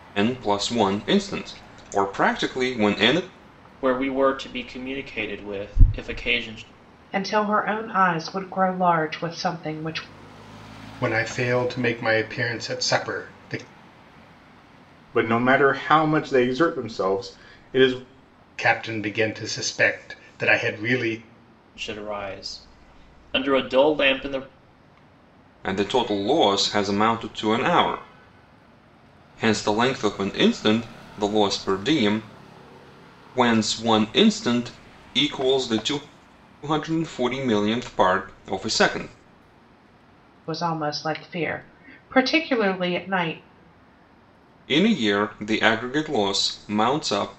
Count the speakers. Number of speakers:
five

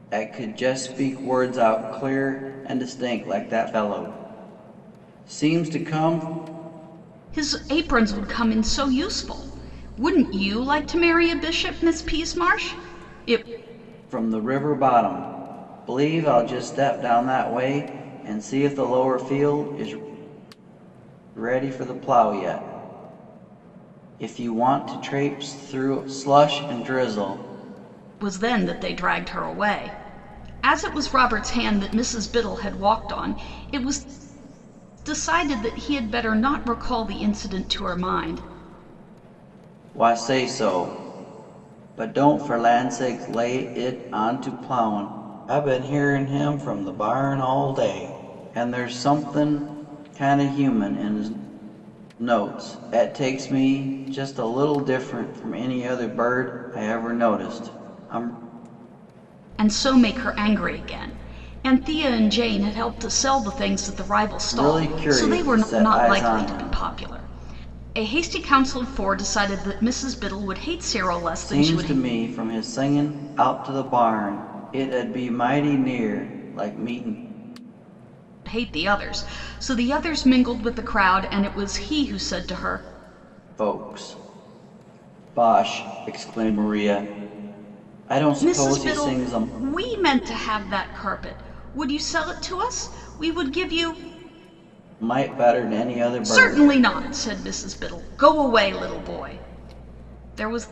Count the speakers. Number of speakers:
two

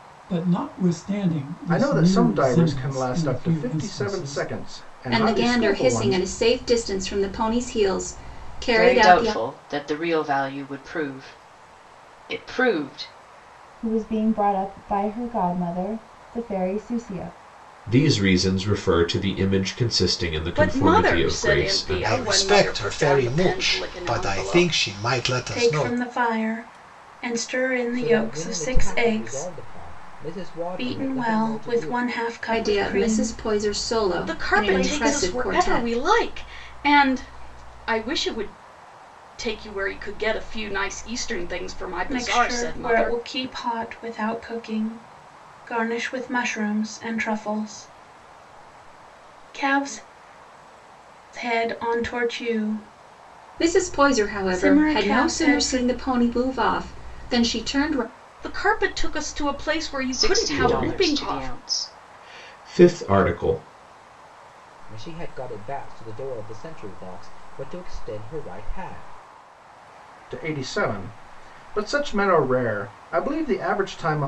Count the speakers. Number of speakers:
ten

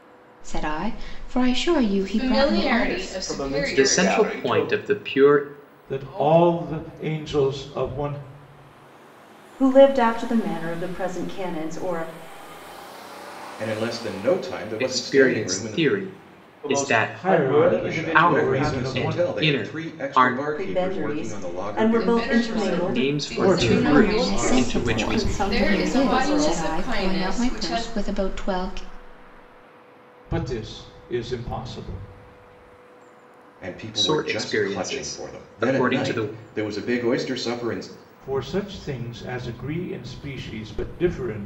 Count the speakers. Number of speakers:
seven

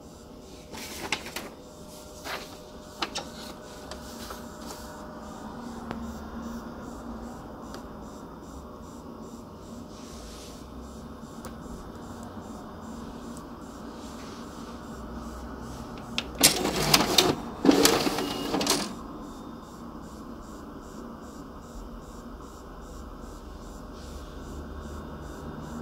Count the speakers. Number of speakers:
zero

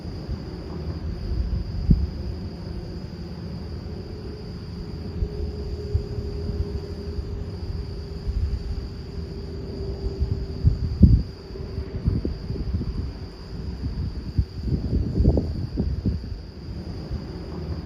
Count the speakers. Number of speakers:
zero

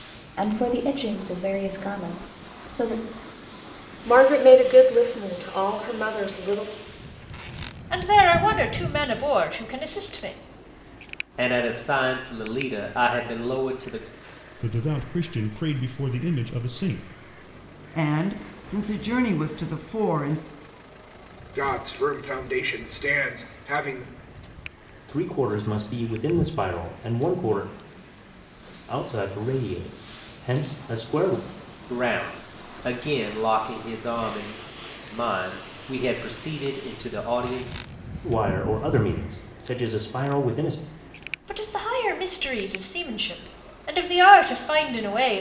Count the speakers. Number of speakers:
eight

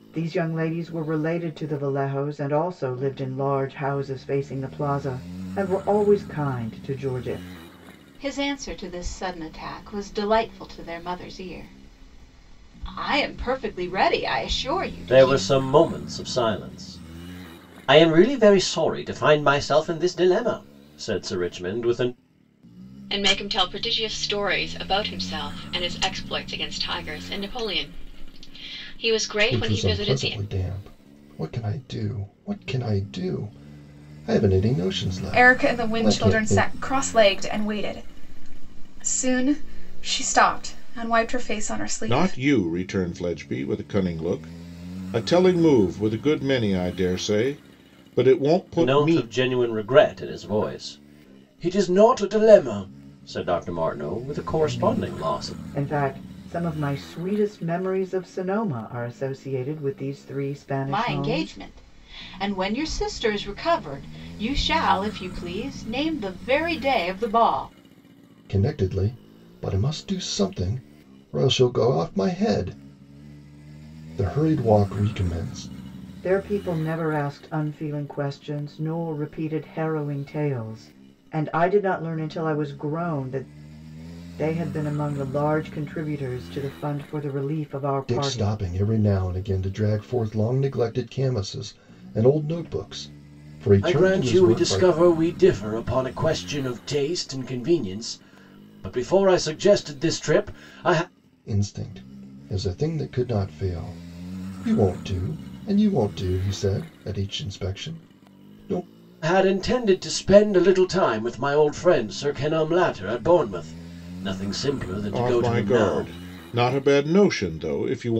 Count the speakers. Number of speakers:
seven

